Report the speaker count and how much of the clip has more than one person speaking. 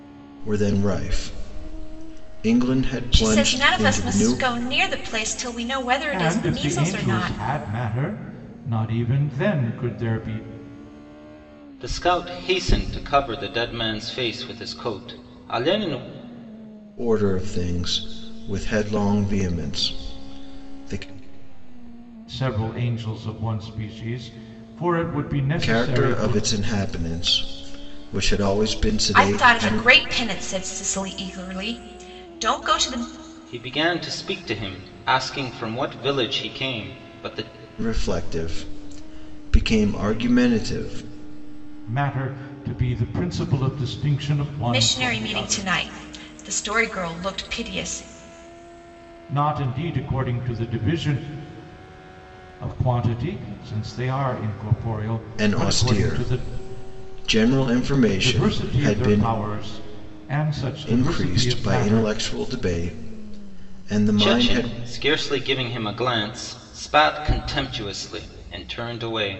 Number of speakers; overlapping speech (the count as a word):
four, about 13%